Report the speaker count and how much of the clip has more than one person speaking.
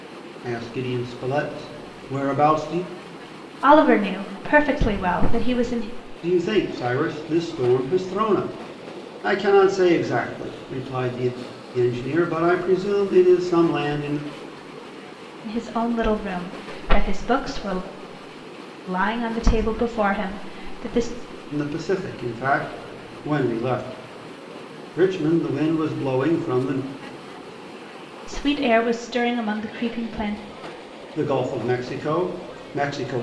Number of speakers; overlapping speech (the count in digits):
2, no overlap